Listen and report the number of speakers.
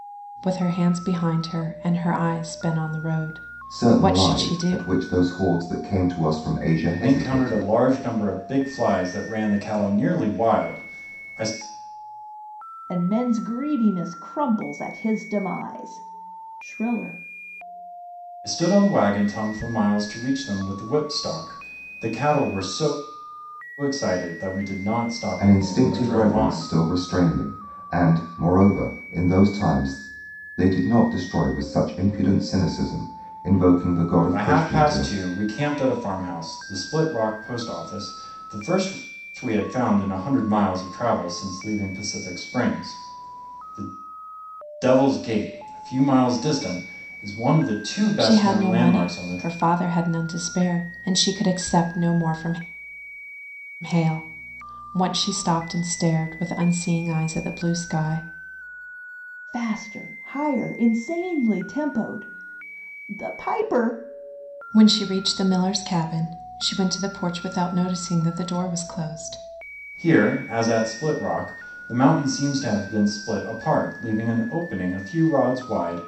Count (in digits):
4